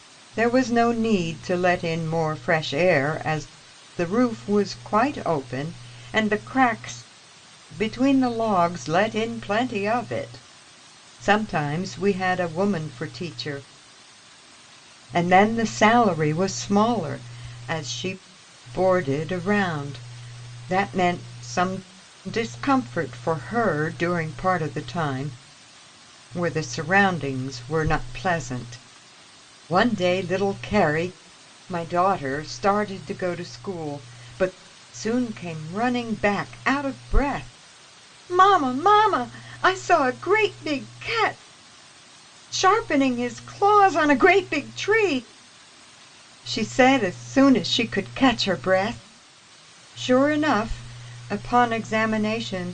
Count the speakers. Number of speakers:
1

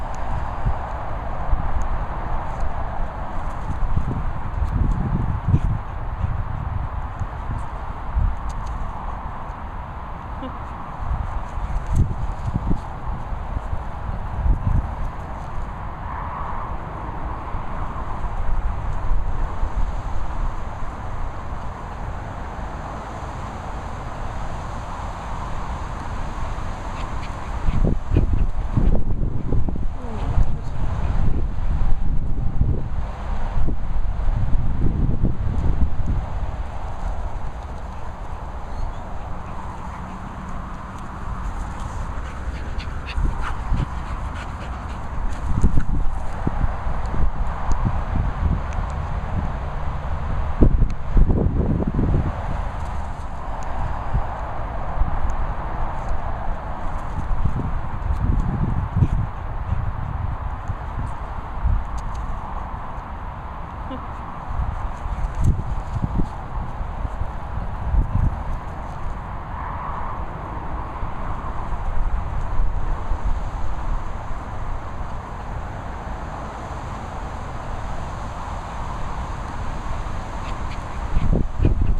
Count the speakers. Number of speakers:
0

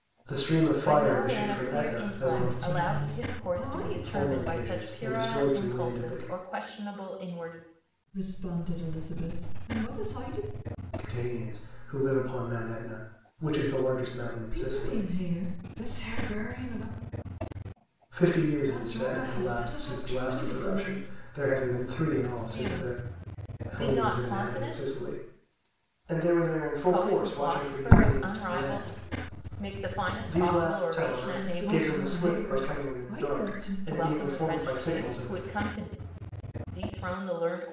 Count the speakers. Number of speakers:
3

